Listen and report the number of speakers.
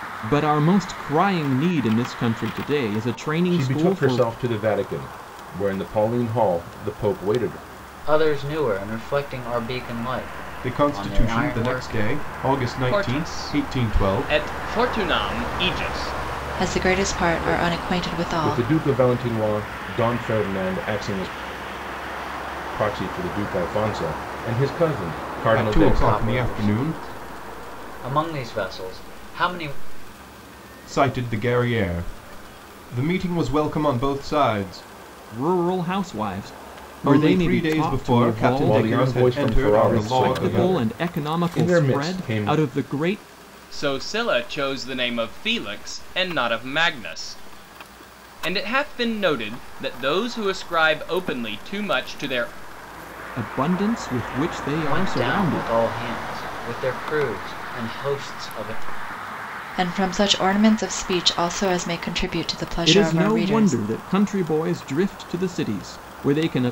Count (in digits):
6